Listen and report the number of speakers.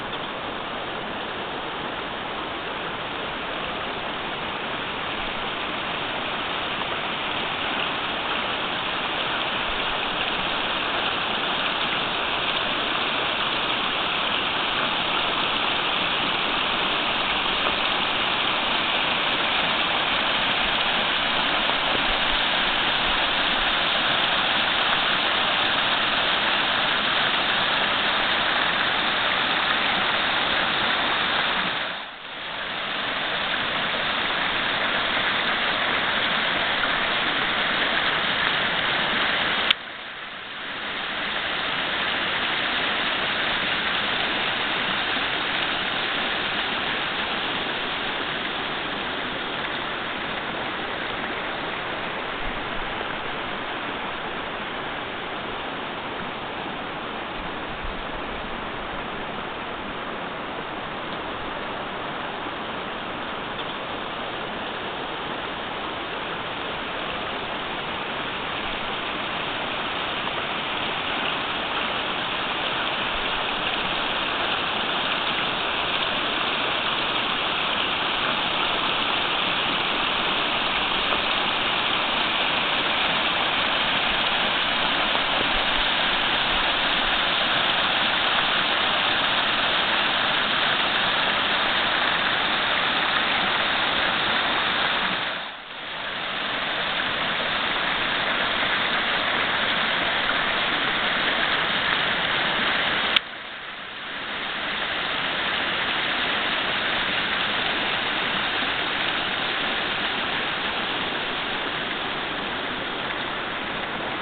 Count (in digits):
0